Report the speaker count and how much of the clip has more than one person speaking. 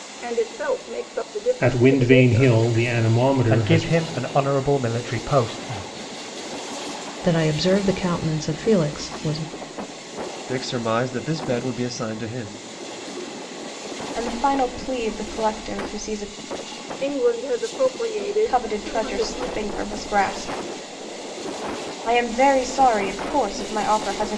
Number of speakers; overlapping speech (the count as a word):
six, about 10%